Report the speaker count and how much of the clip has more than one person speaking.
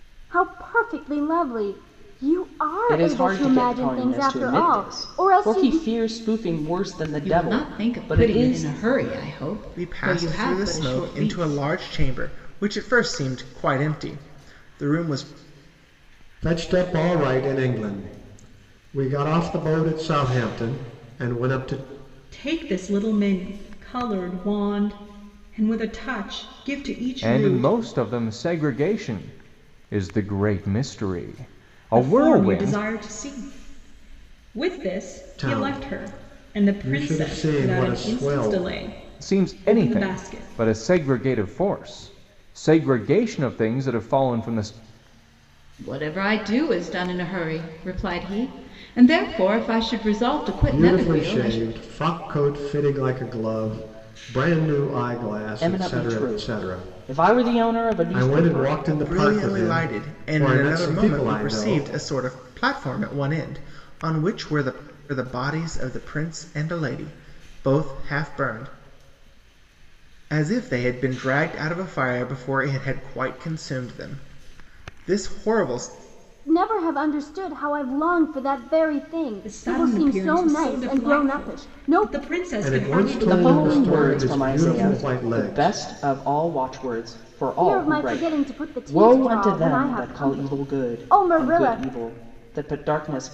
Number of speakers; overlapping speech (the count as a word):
seven, about 31%